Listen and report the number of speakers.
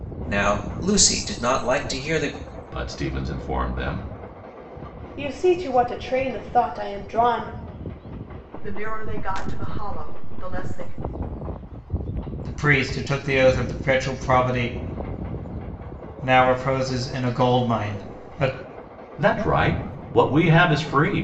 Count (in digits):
5